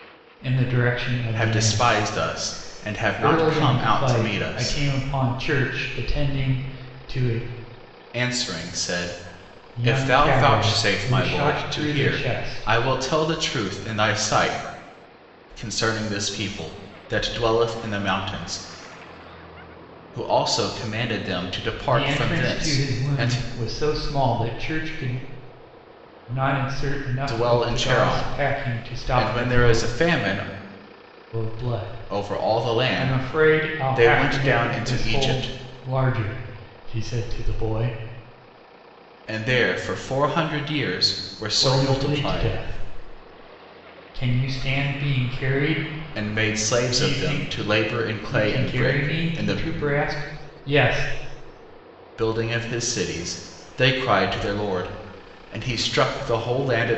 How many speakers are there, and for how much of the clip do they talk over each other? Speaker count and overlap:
two, about 32%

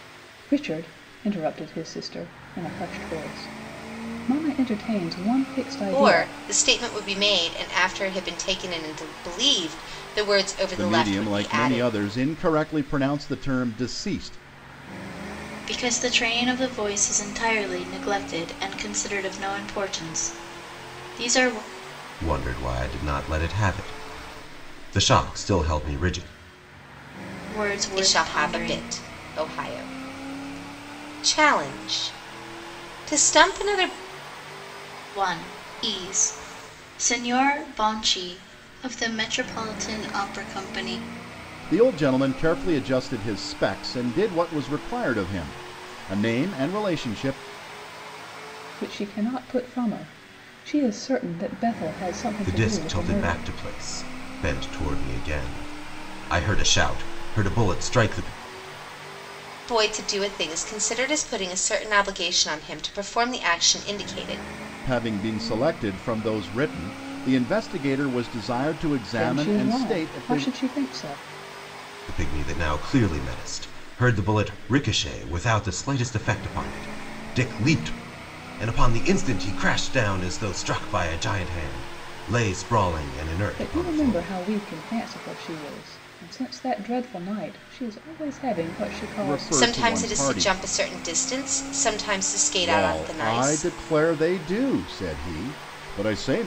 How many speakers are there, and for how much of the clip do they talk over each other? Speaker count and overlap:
five, about 9%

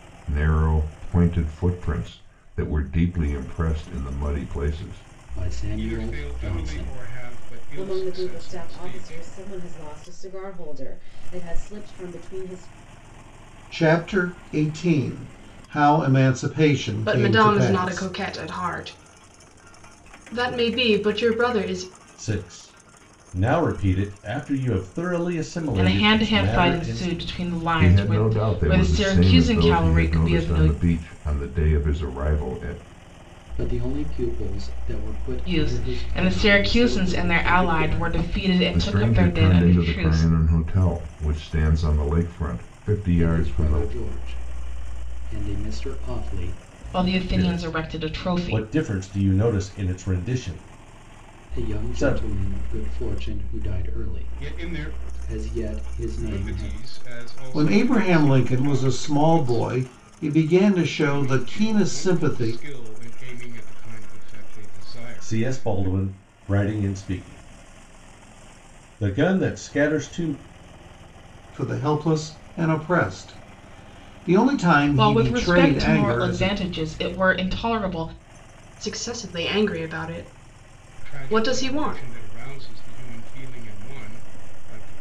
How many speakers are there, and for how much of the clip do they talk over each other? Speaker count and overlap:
eight, about 30%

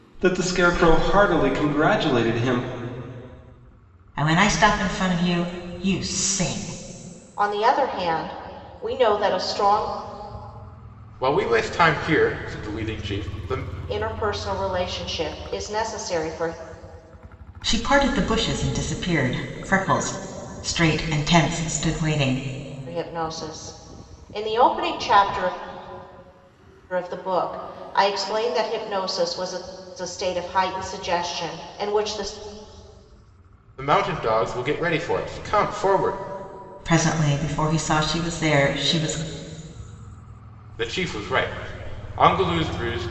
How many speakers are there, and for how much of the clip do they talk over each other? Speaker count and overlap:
four, no overlap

